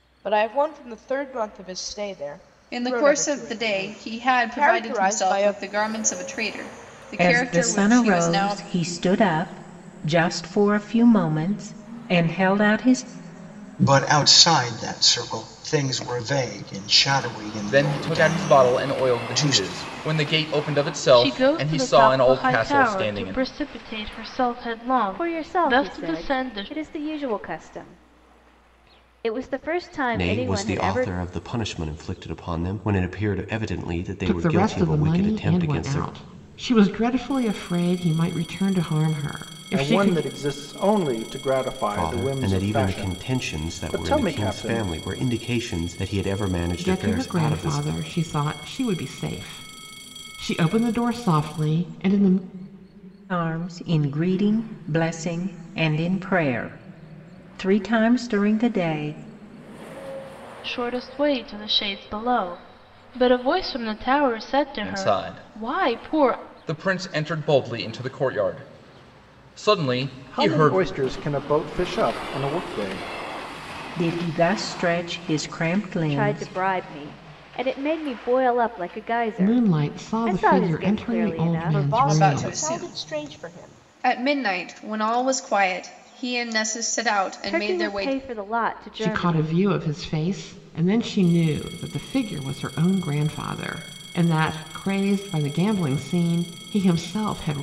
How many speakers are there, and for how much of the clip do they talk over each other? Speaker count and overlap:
10, about 27%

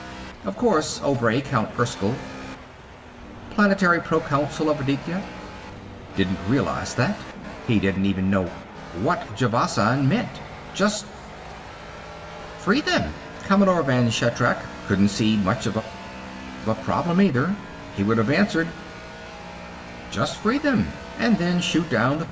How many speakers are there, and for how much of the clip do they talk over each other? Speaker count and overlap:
1, no overlap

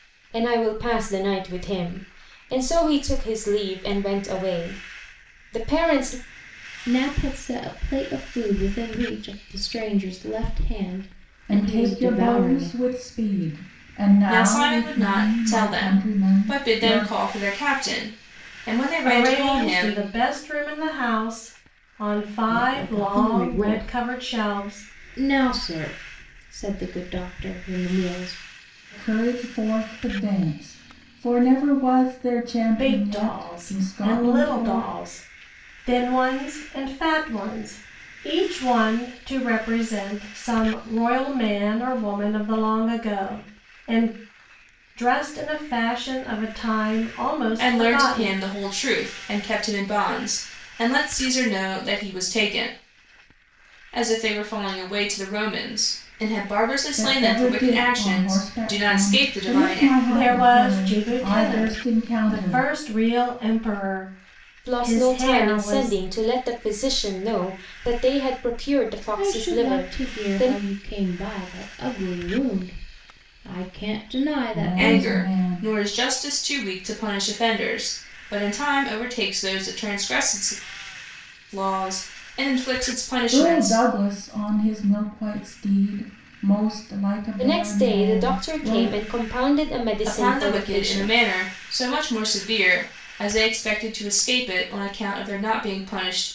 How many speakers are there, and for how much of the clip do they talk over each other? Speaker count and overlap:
5, about 24%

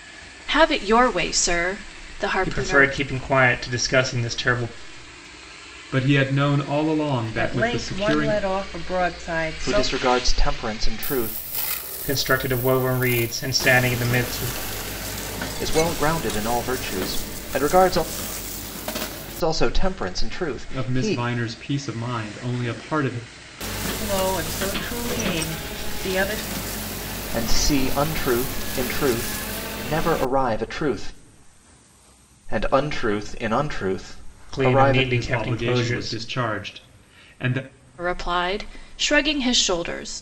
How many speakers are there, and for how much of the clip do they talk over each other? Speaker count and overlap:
5, about 10%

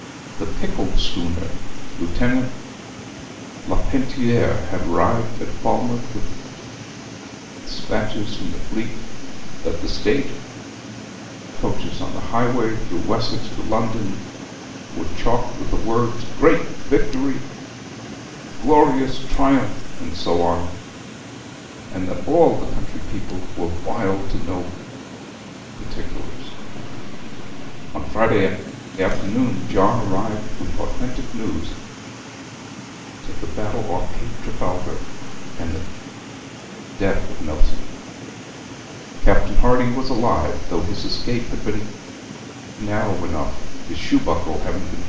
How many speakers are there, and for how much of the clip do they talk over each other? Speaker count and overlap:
1, no overlap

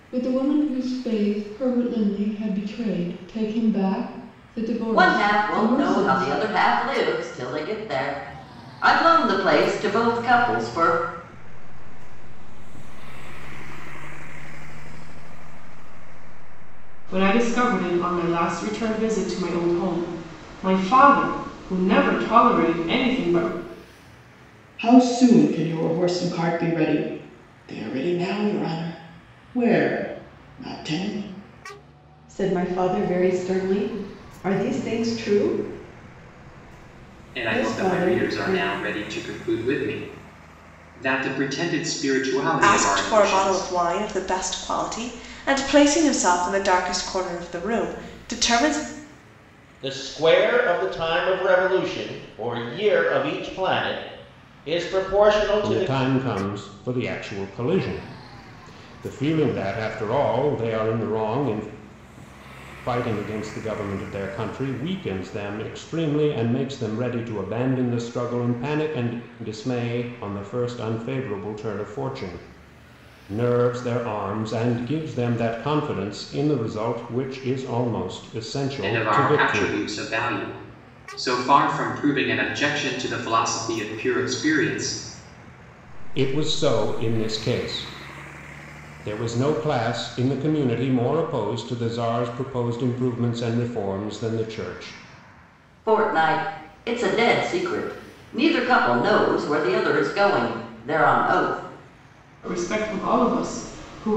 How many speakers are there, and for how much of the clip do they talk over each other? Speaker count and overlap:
10, about 7%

